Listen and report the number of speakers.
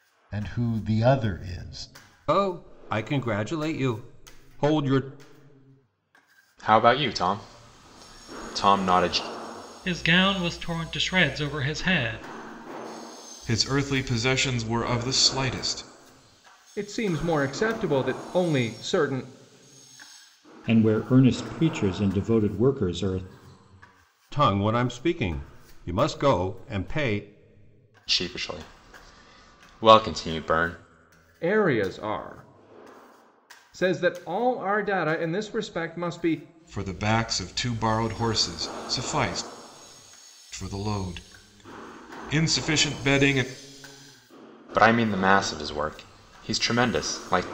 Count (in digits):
7